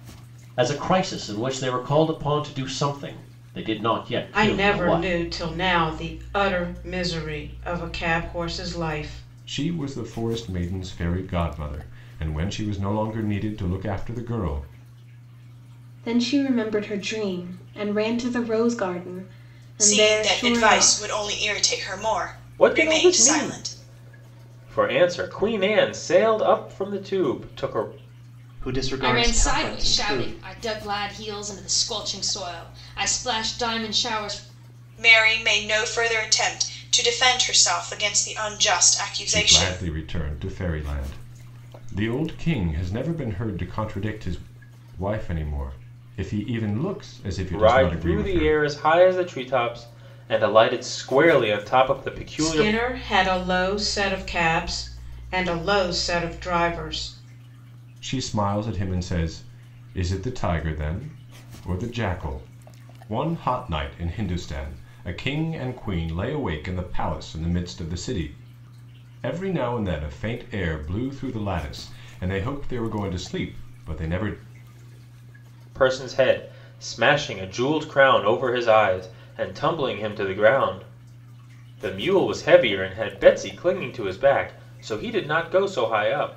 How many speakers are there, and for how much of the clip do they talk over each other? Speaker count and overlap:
eight, about 8%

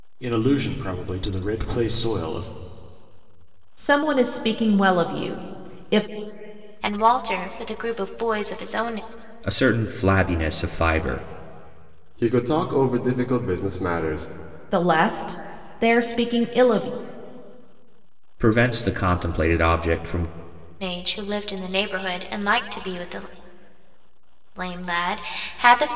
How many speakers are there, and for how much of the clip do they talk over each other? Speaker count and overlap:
five, no overlap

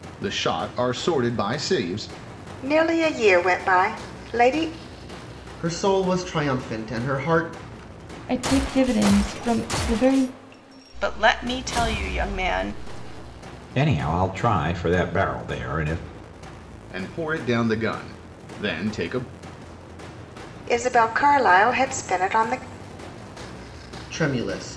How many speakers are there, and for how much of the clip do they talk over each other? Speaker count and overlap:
six, no overlap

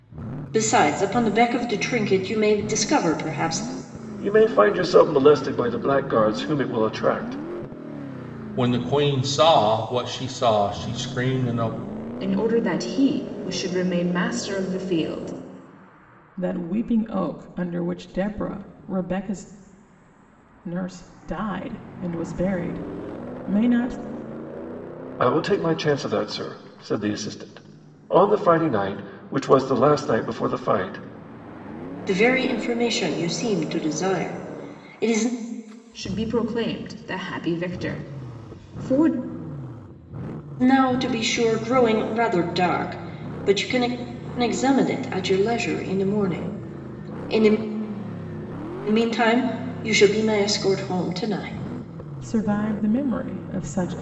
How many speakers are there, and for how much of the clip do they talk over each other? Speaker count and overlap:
five, no overlap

